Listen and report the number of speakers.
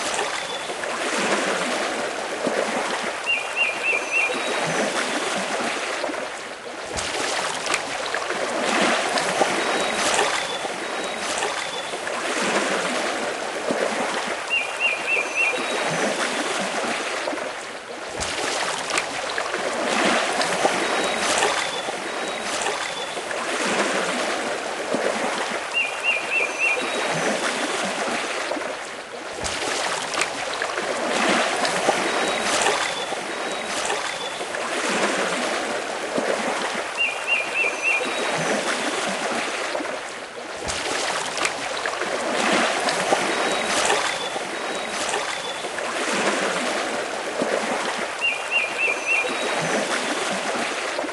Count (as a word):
zero